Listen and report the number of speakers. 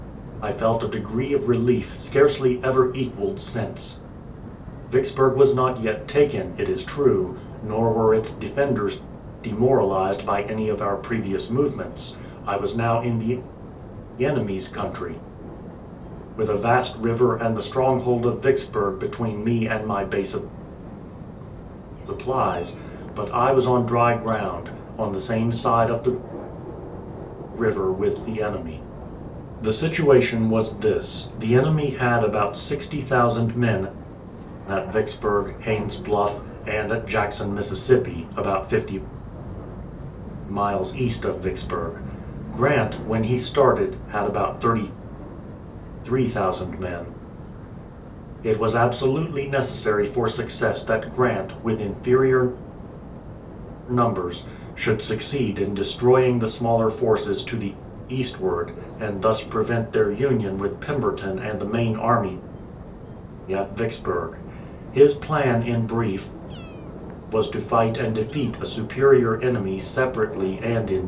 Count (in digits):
1